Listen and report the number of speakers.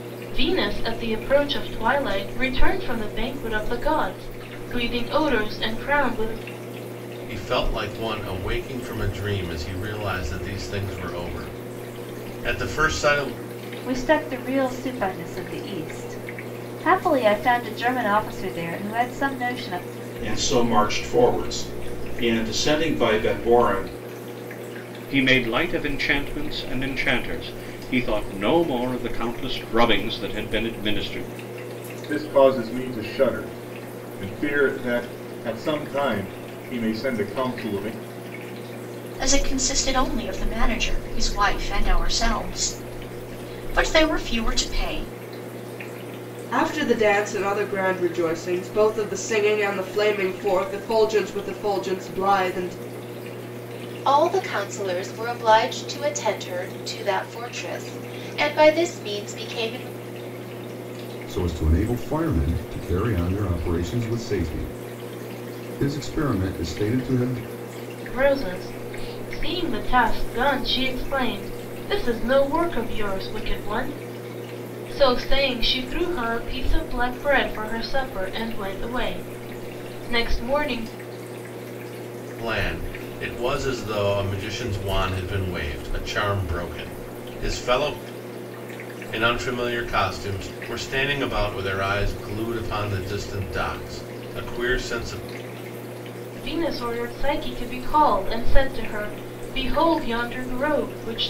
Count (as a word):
ten